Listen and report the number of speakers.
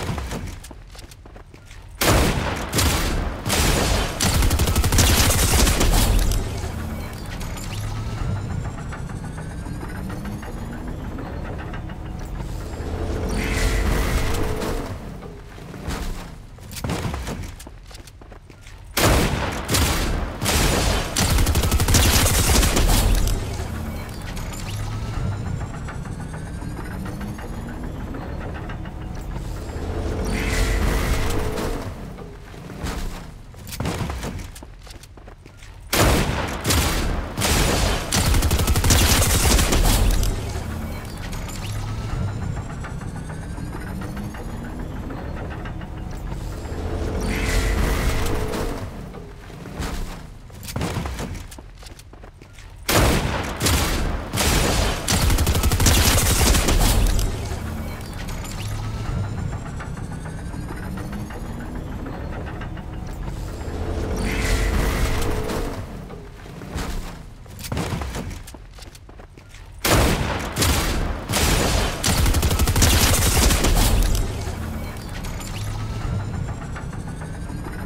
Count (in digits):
0